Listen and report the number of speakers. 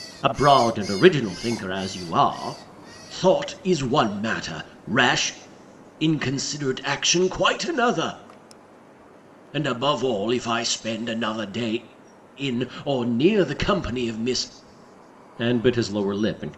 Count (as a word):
one